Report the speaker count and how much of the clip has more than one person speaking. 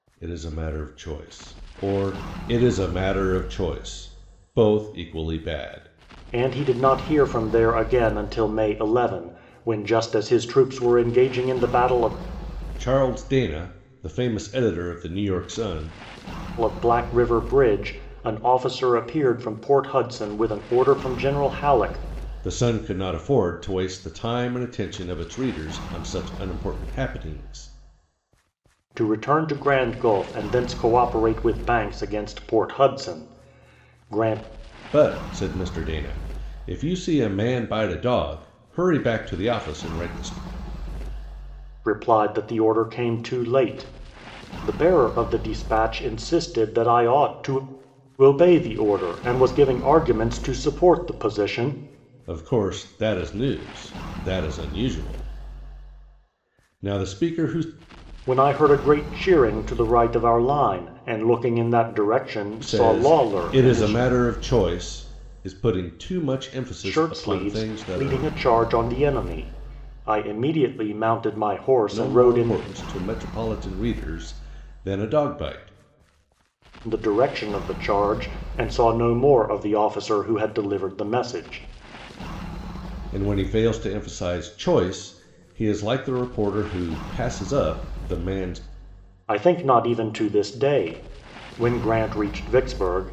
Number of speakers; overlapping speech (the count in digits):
2, about 4%